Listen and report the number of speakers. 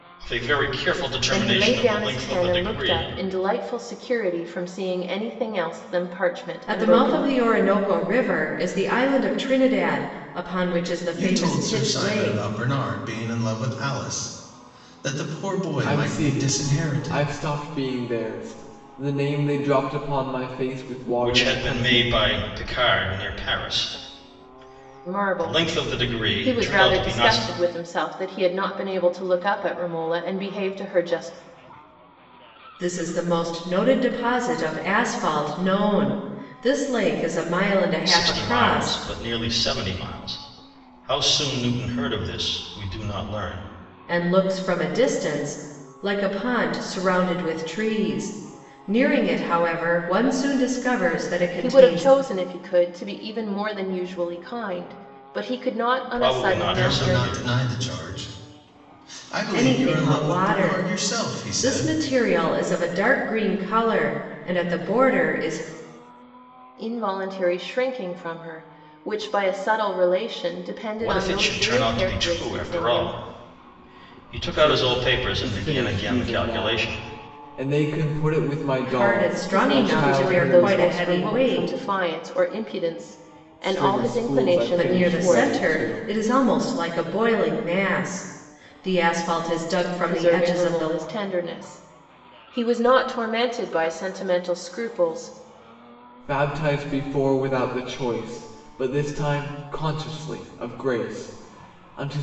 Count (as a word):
five